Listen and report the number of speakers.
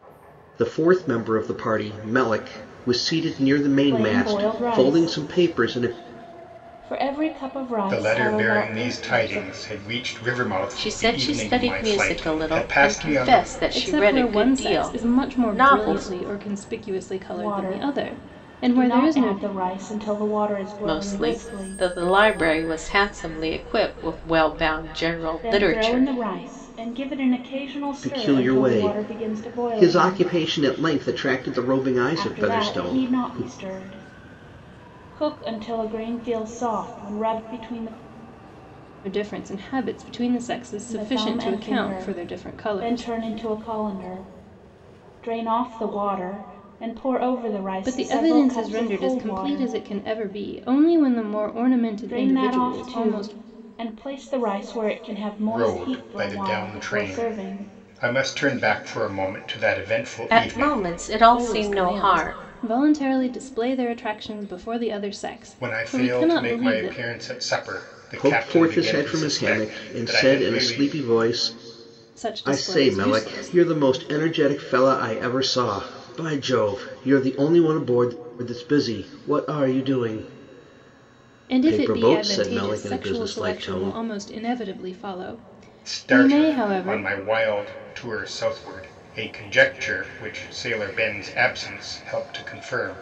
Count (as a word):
five